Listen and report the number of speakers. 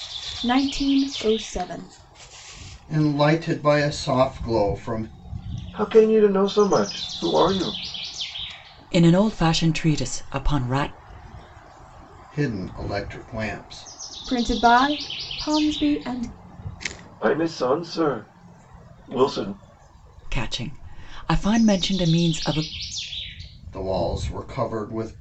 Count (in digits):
4